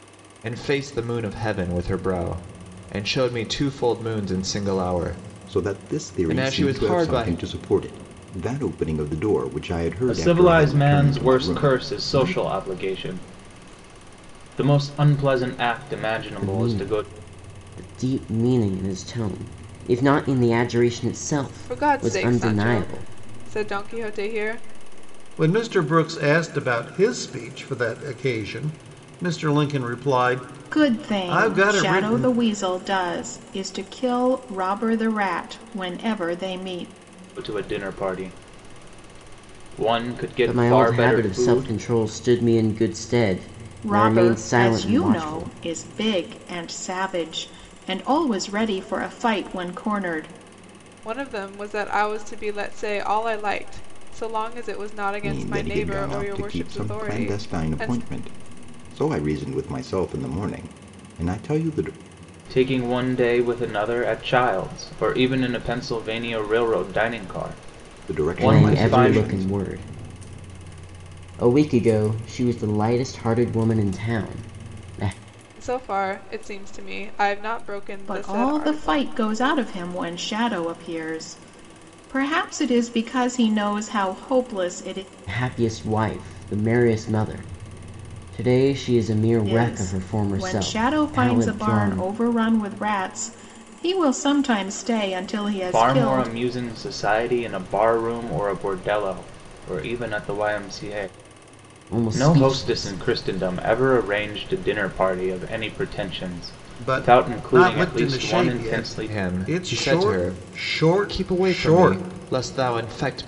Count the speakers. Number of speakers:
seven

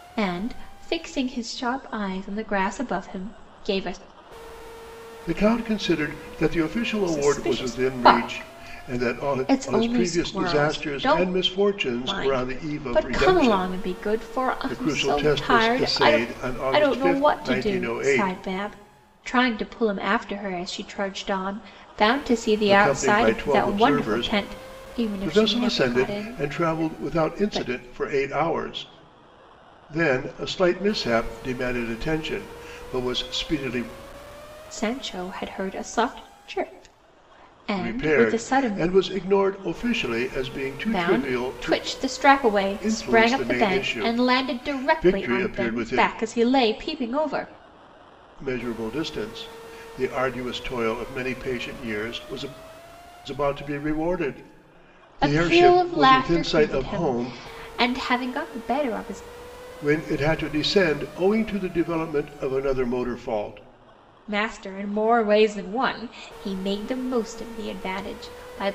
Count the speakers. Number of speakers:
two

